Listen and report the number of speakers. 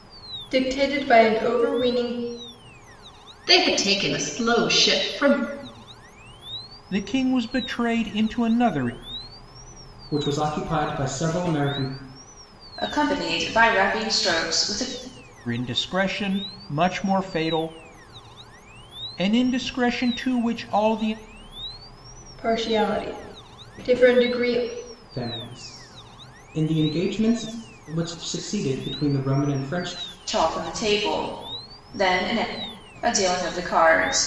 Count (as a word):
five